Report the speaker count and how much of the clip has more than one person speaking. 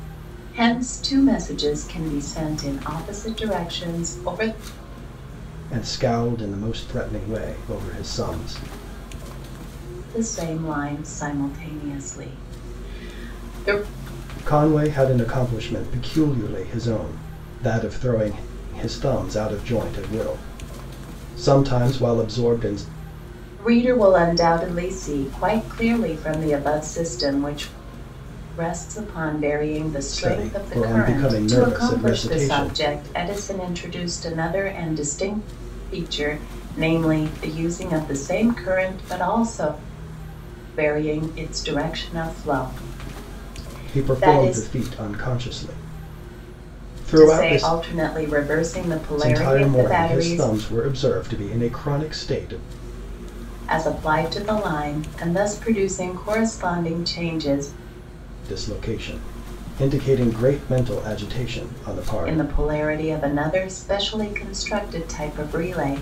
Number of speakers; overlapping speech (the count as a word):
two, about 9%